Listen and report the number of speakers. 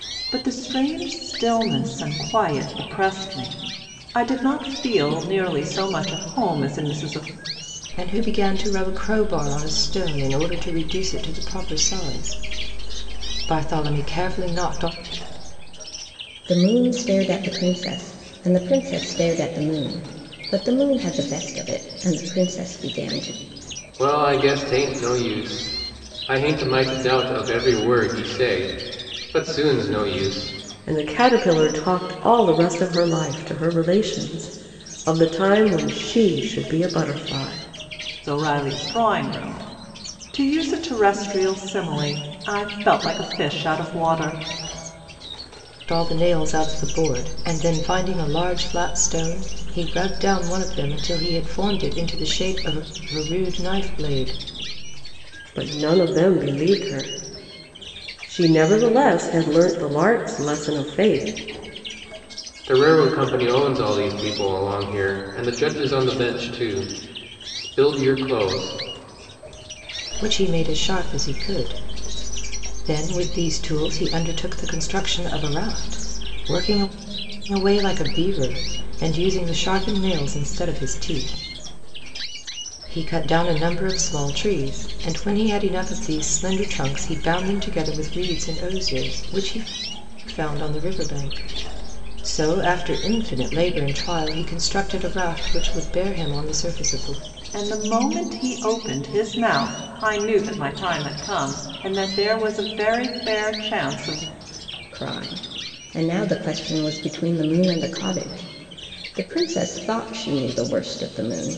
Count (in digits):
5